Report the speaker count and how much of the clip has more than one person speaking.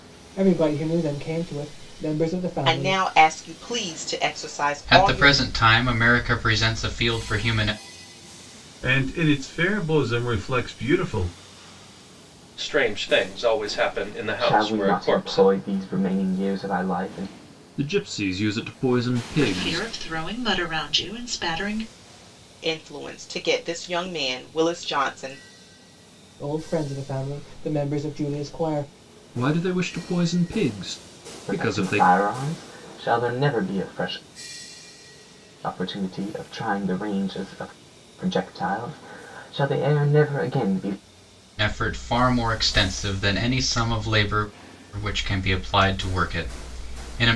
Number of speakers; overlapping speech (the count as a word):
eight, about 7%